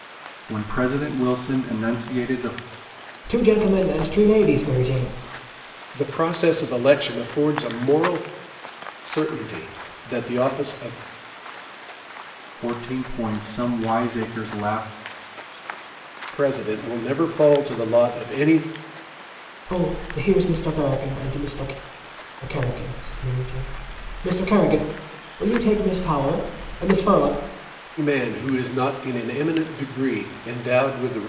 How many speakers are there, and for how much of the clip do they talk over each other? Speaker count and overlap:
three, no overlap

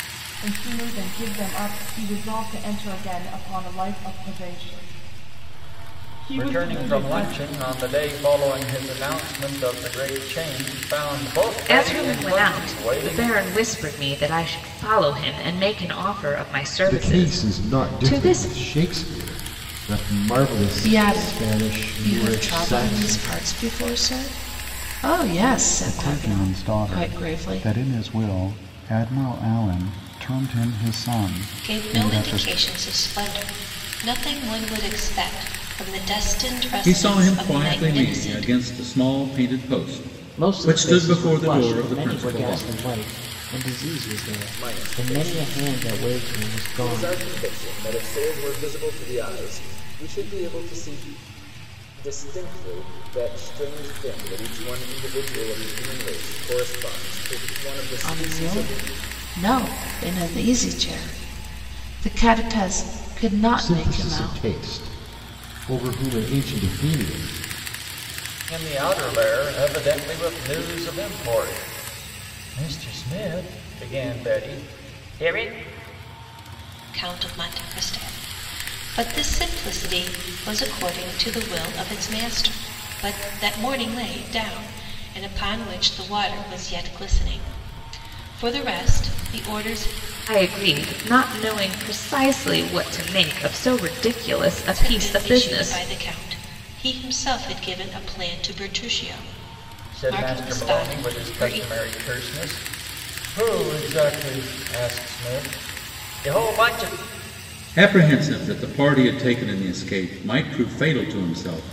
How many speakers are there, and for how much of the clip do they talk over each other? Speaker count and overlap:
ten, about 19%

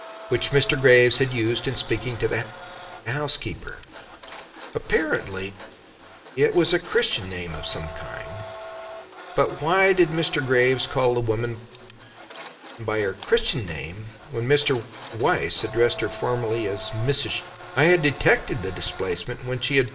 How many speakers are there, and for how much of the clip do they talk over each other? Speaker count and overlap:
one, no overlap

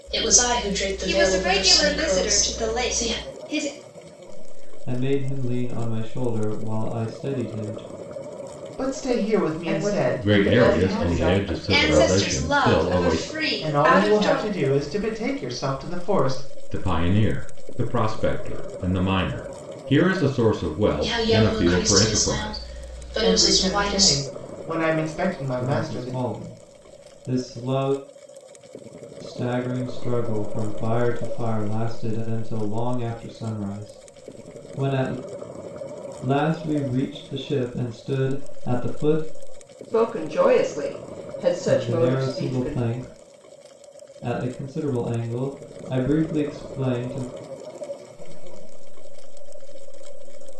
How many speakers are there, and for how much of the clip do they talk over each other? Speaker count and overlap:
seven, about 40%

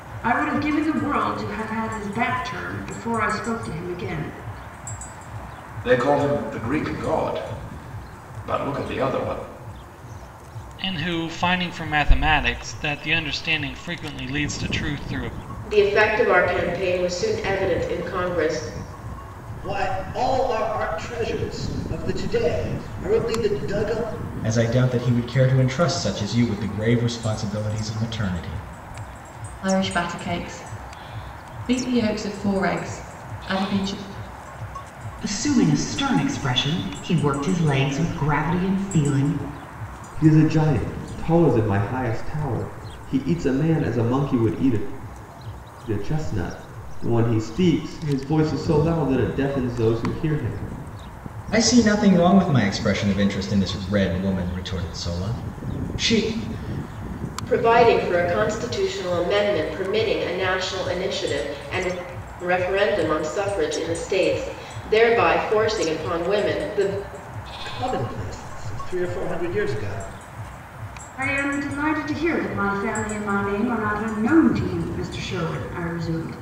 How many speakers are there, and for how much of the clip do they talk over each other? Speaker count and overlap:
nine, no overlap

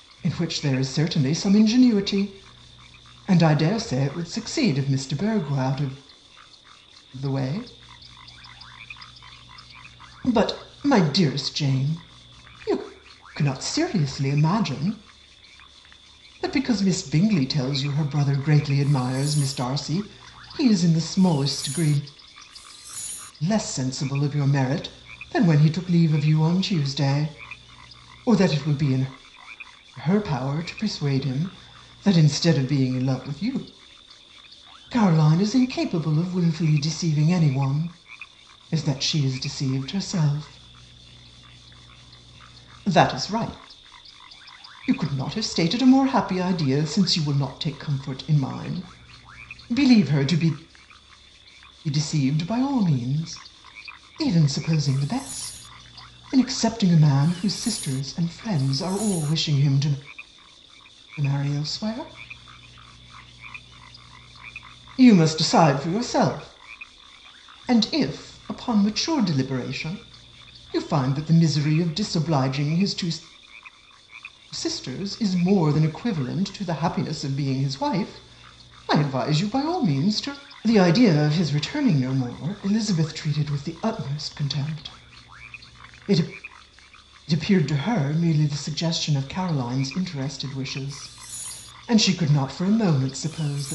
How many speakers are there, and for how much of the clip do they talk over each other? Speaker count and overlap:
one, no overlap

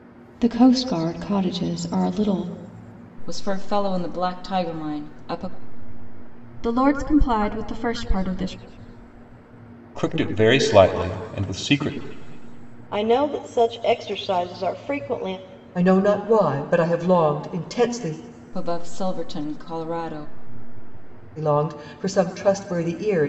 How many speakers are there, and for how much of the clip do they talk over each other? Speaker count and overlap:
six, no overlap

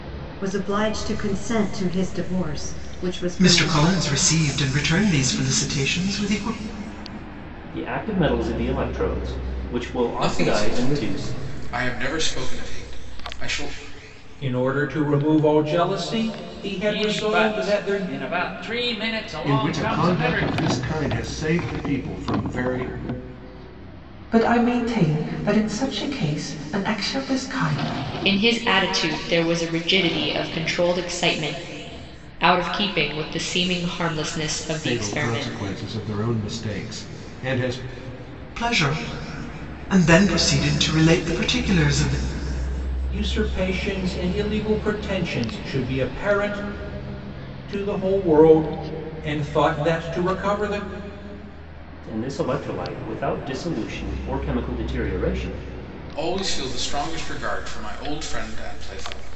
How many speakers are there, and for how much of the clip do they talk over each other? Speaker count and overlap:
nine, about 9%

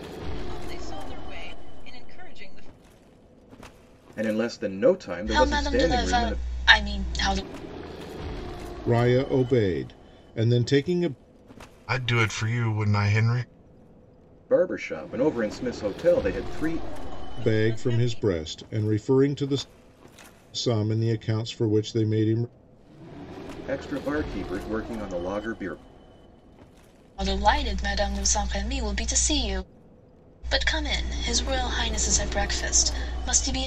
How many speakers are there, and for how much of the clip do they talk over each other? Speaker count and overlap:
five, about 7%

